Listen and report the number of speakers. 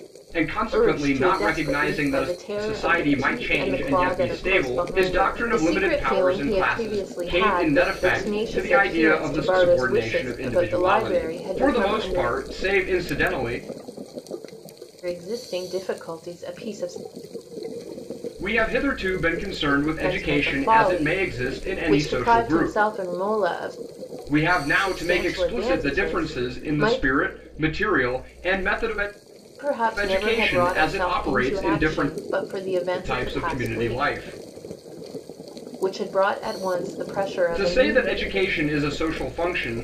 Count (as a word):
two